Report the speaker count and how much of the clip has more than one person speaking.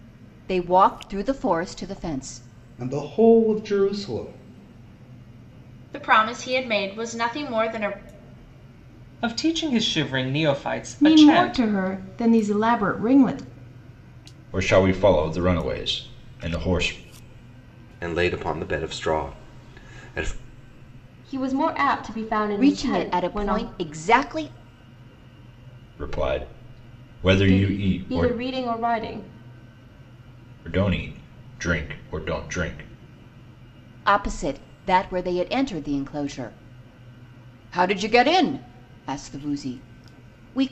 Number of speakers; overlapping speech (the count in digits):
8, about 7%